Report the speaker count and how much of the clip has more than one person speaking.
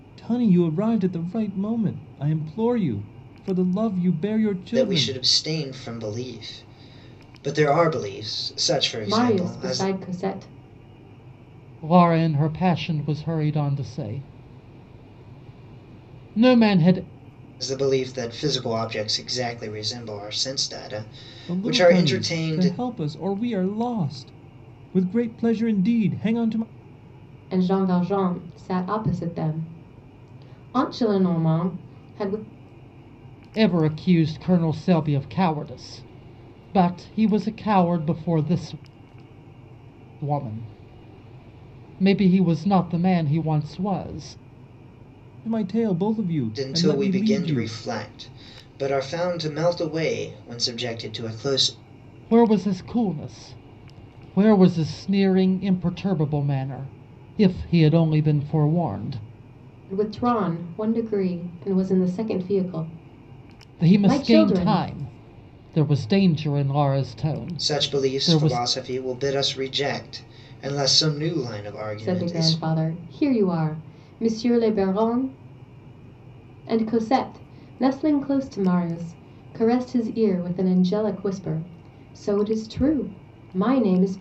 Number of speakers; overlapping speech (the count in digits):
4, about 8%